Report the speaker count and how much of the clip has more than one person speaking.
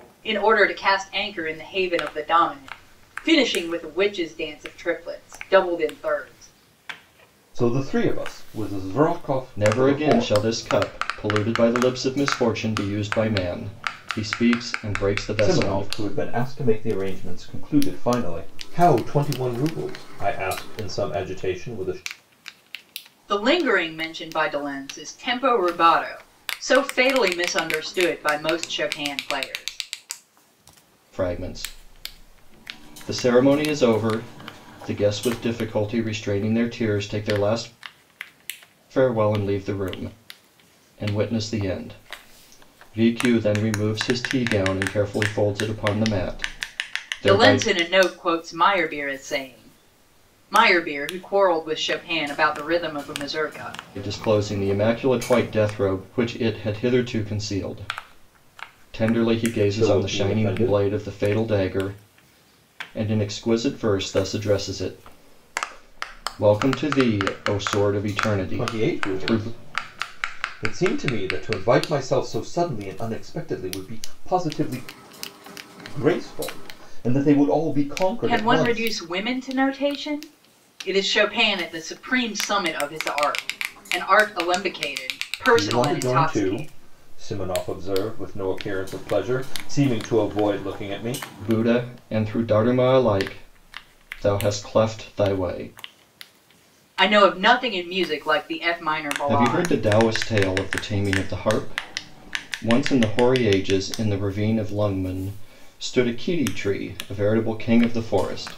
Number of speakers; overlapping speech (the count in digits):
3, about 6%